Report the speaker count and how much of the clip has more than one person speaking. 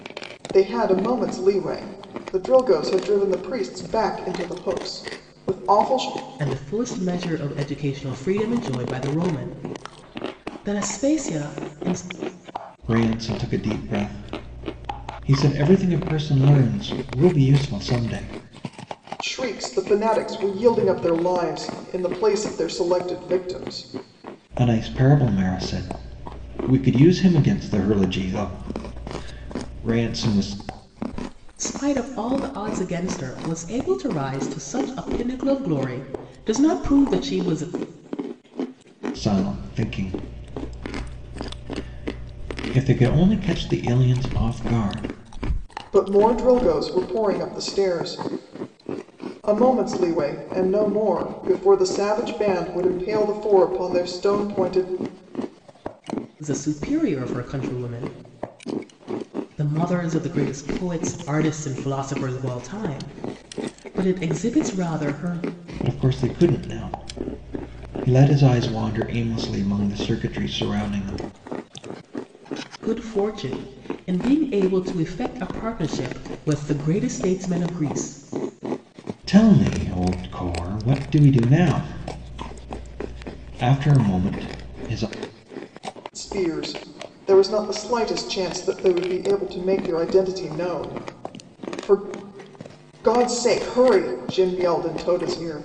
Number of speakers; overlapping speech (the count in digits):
3, no overlap